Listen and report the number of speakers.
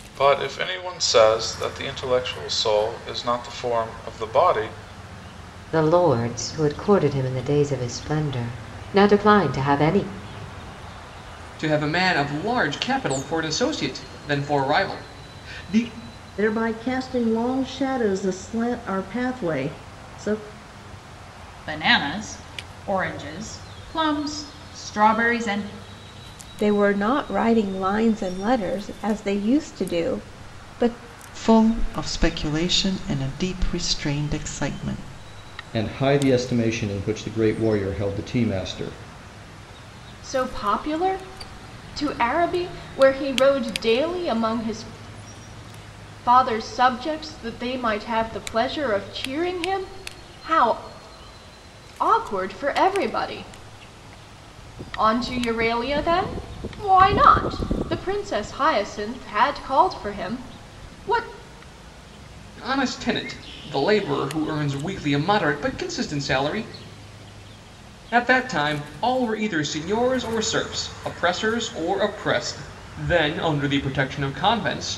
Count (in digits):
9